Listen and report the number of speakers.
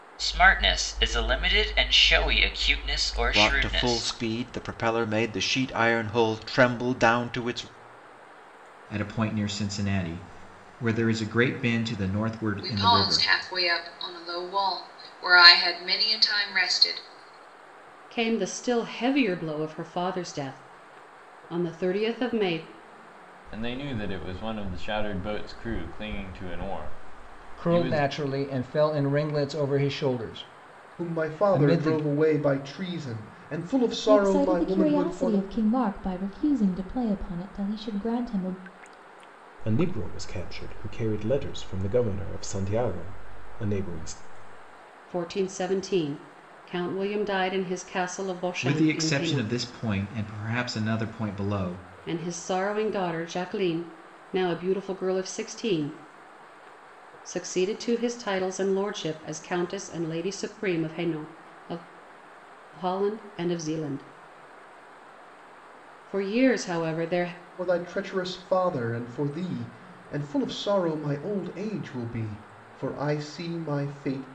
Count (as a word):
ten